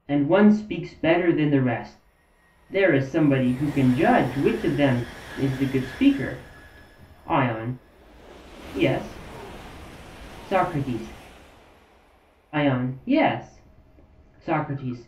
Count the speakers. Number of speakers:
1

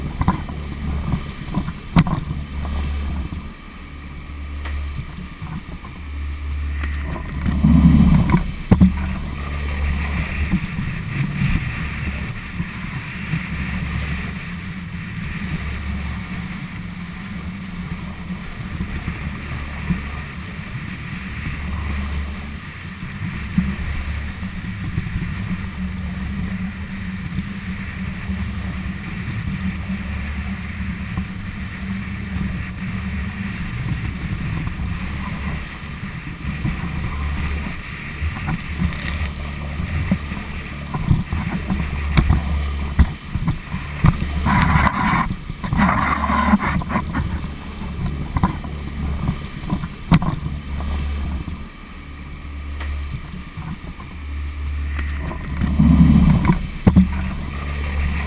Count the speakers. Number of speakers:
0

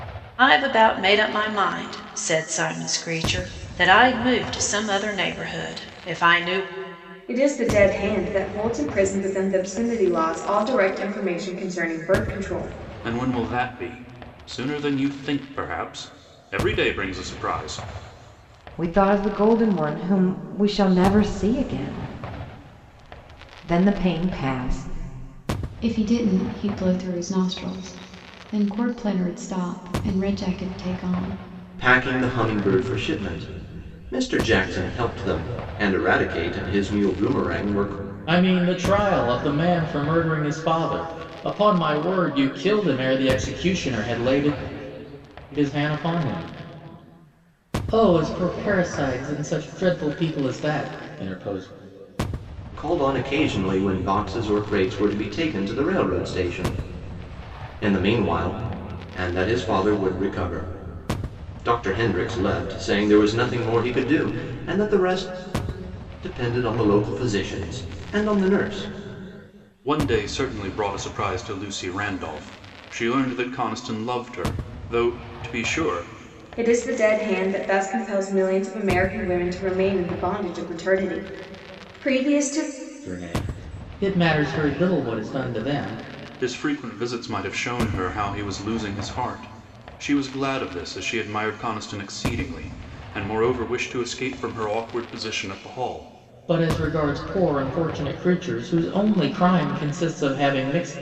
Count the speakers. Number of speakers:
7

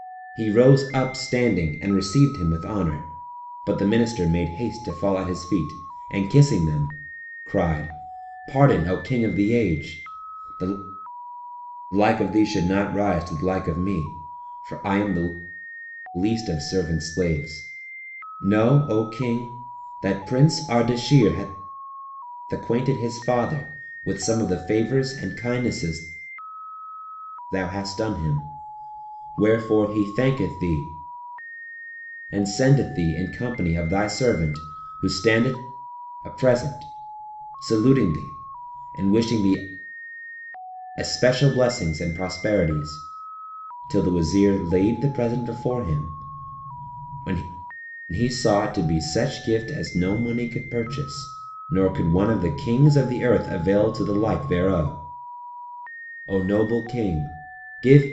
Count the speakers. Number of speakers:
1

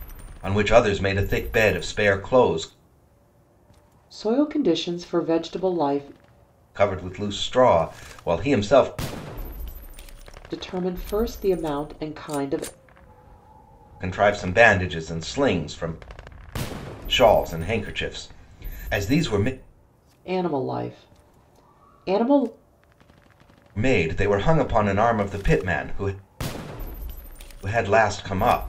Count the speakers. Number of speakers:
2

